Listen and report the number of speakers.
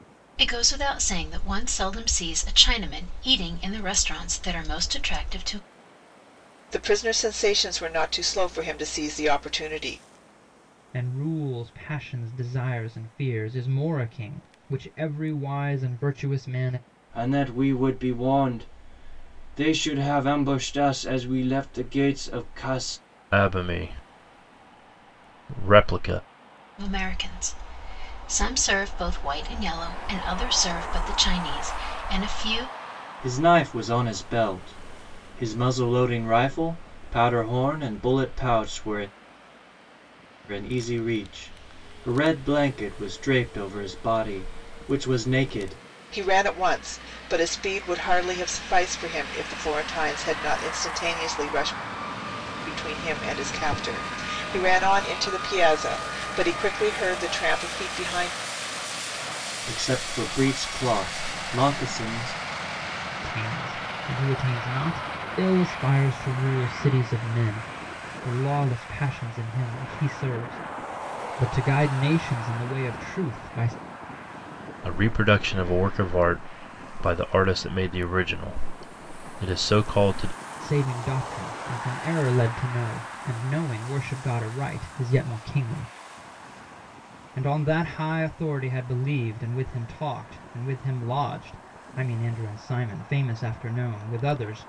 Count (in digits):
5